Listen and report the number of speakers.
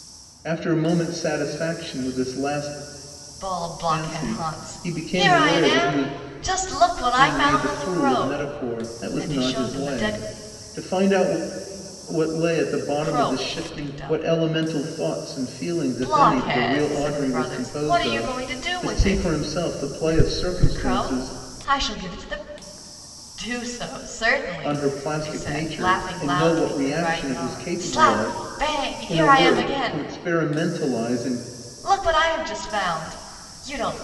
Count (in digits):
2